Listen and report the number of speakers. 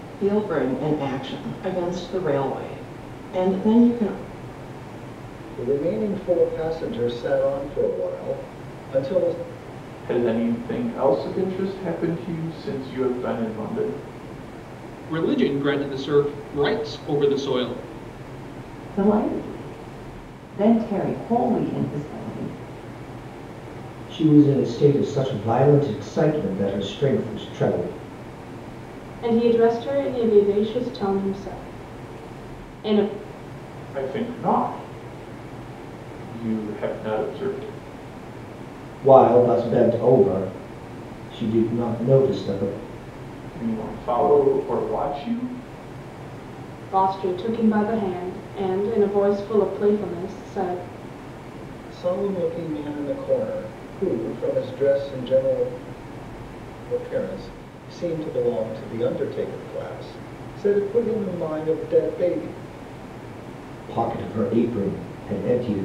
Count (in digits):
7